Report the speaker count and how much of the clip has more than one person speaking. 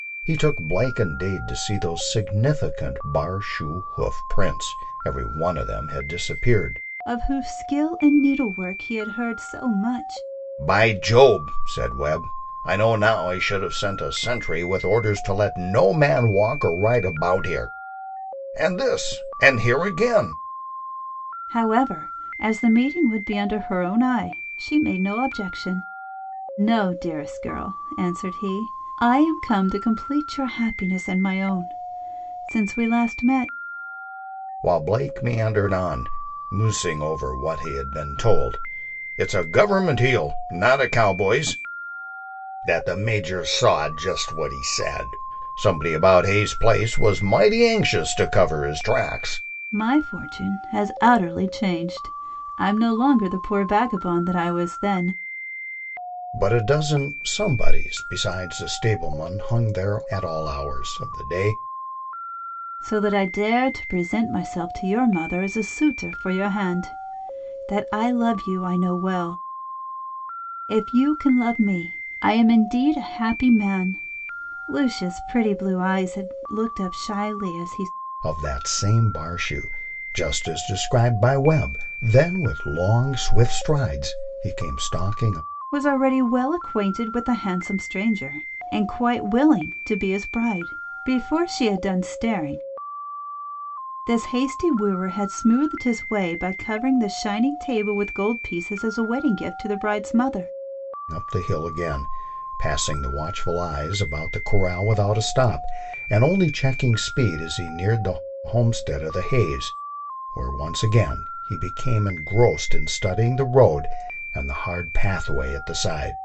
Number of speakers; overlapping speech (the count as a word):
two, no overlap